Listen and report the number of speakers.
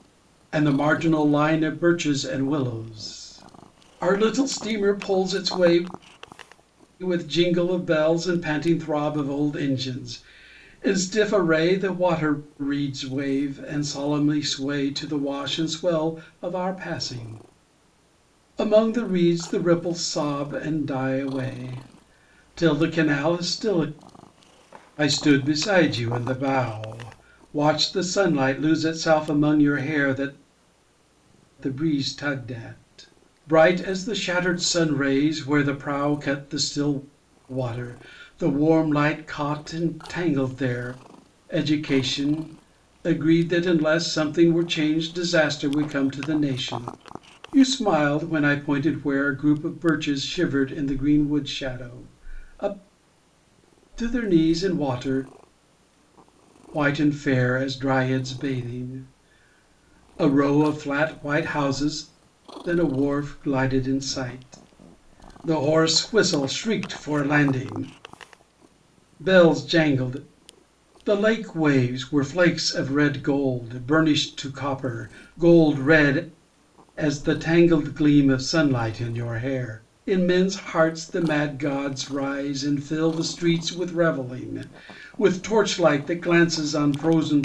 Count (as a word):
one